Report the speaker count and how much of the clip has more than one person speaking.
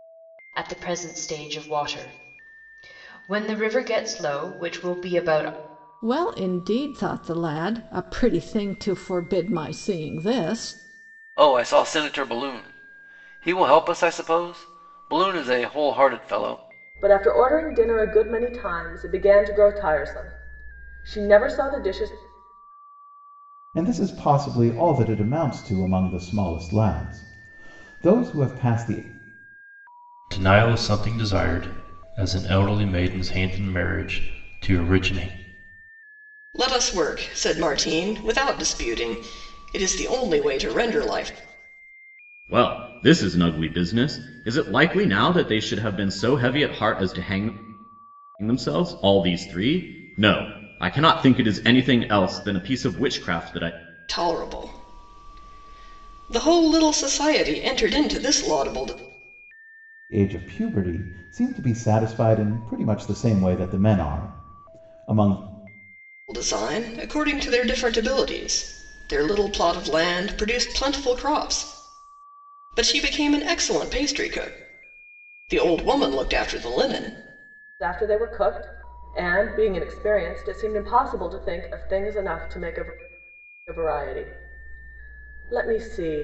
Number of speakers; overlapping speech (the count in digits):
8, no overlap